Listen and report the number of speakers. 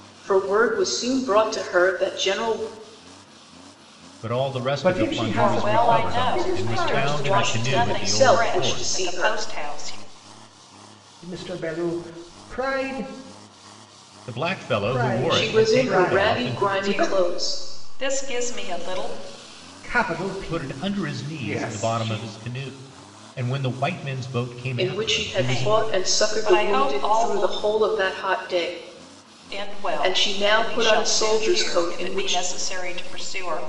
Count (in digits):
4